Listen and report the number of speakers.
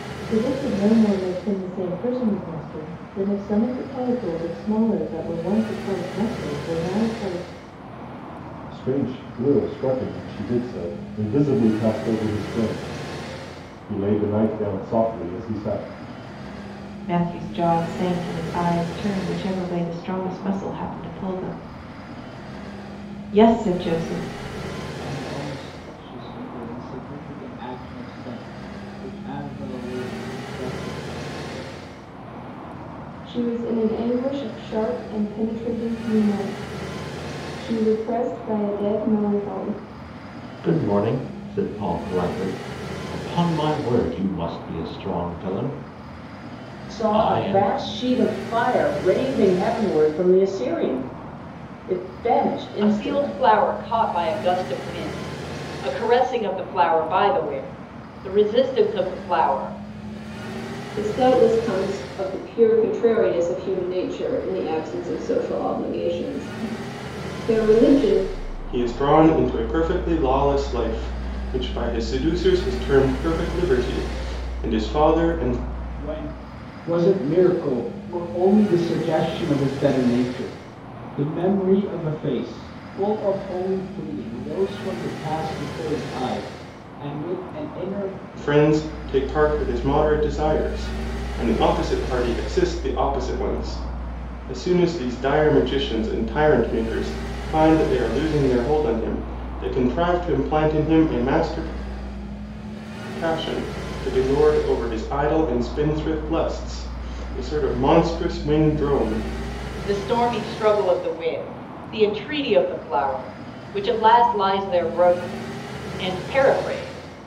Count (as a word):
ten